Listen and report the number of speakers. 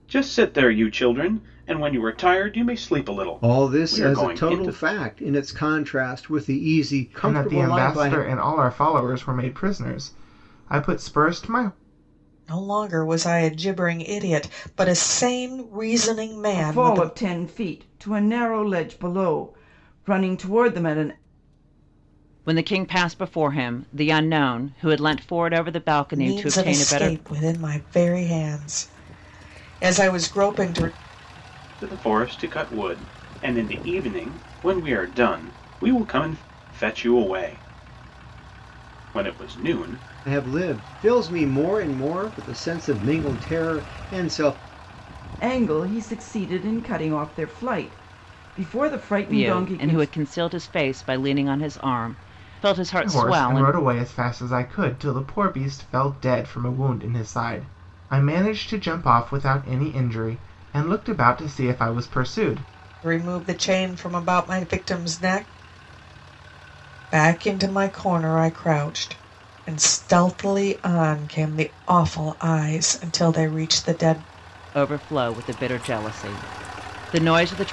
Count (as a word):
six